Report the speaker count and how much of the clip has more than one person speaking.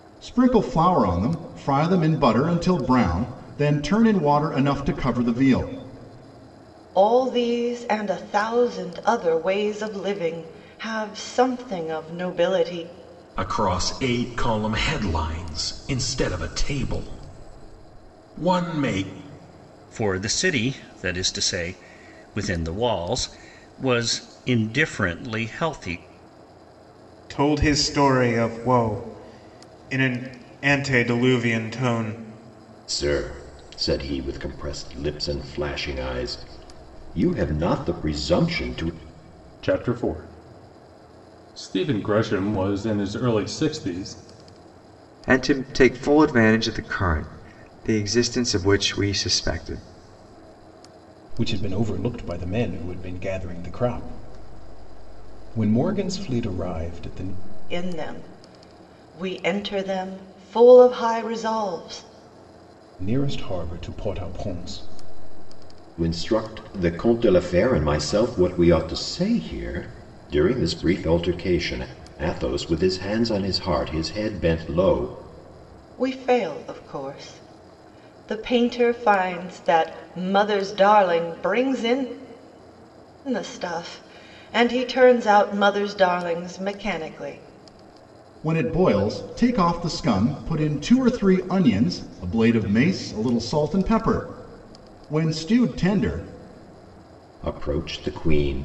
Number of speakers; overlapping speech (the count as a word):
nine, no overlap